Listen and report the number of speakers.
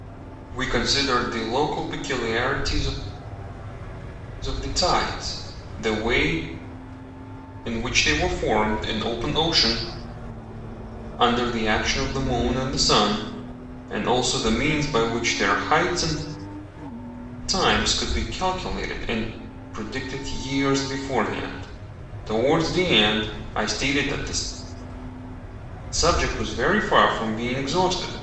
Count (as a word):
one